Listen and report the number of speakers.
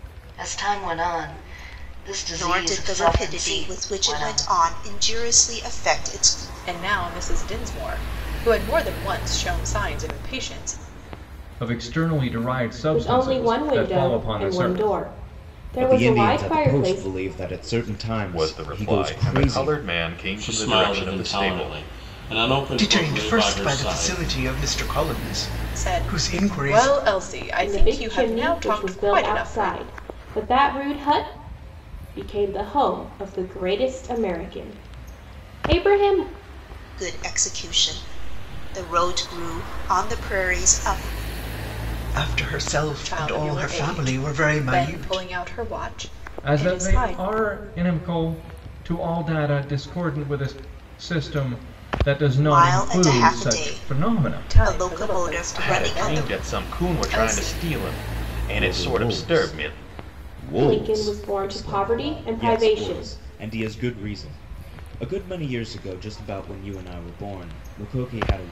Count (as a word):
nine